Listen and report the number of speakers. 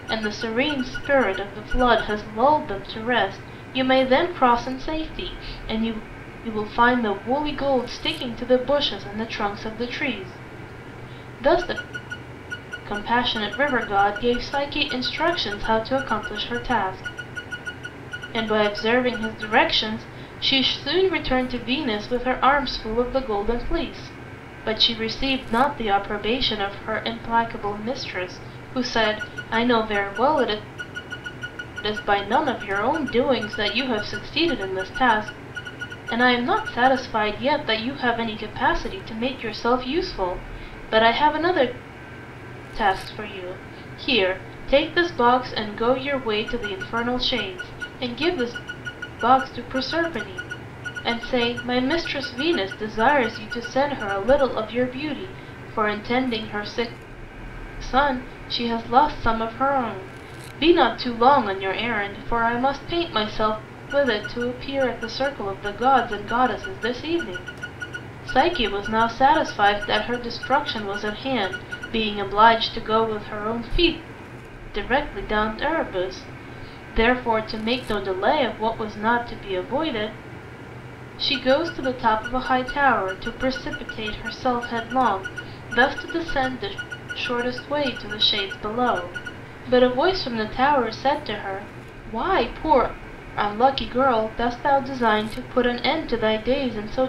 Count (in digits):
1